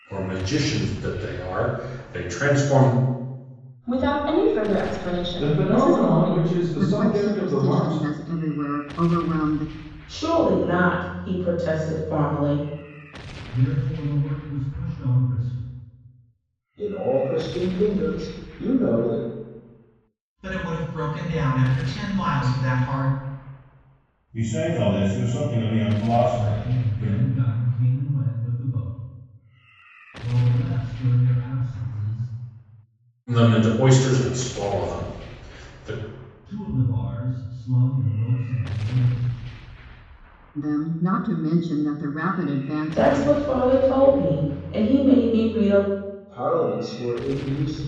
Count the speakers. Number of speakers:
nine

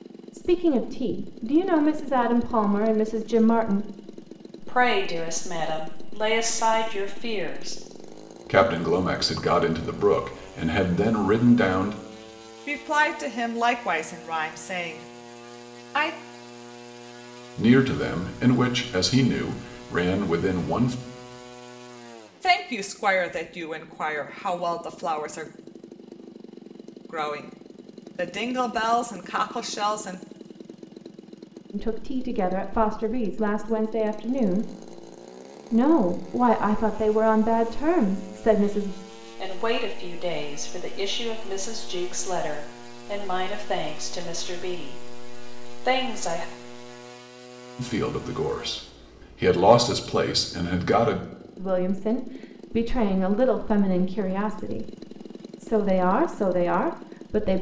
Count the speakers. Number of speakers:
four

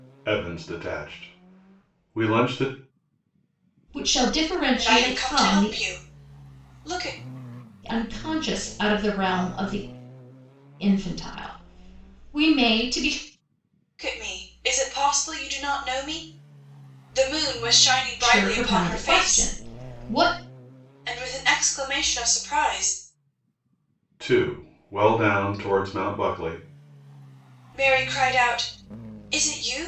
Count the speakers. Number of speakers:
three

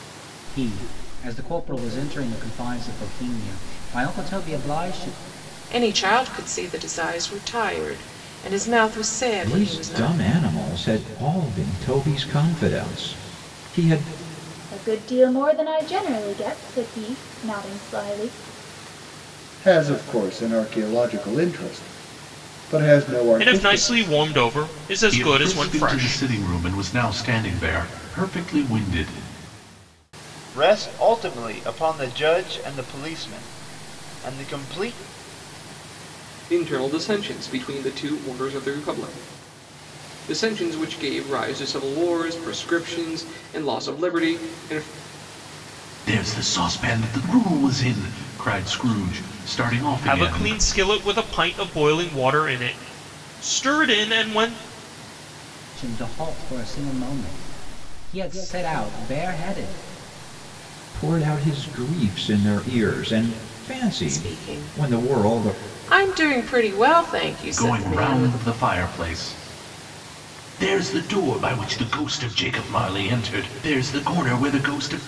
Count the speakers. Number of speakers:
nine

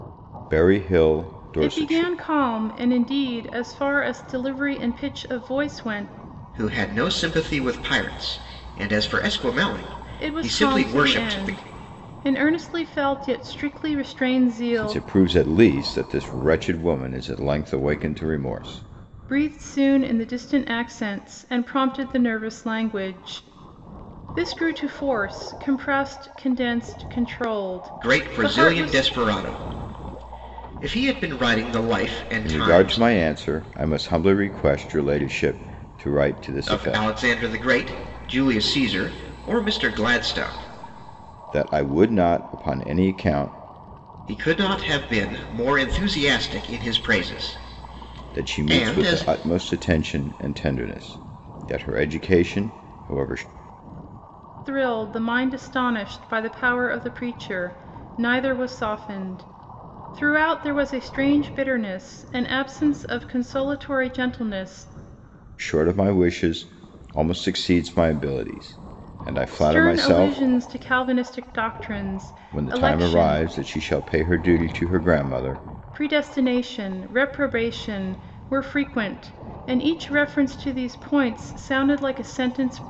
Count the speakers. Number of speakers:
three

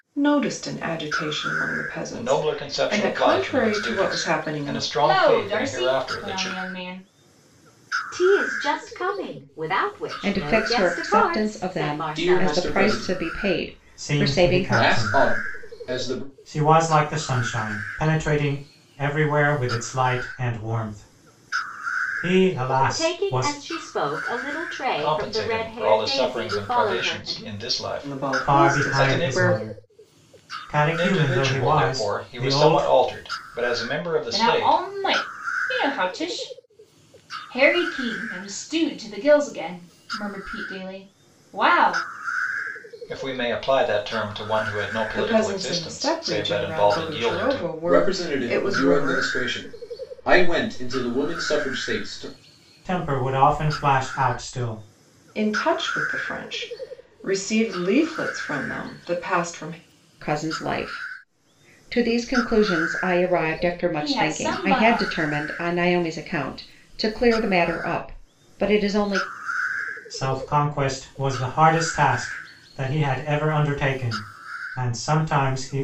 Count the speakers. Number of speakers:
seven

